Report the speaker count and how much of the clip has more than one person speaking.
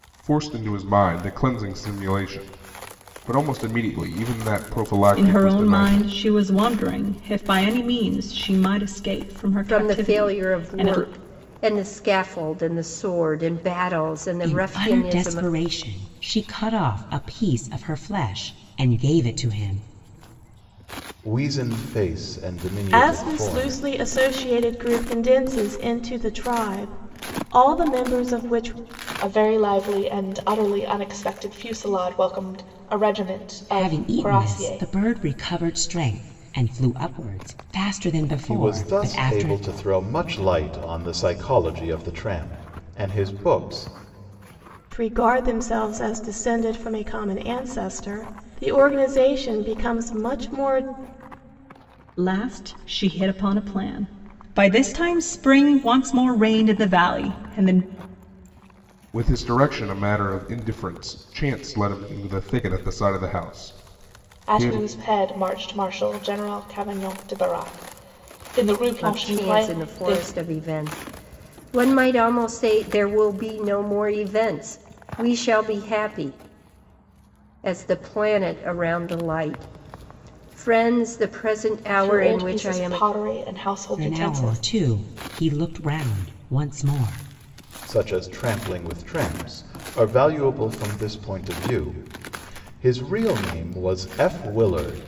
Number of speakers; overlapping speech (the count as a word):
seven, about 11%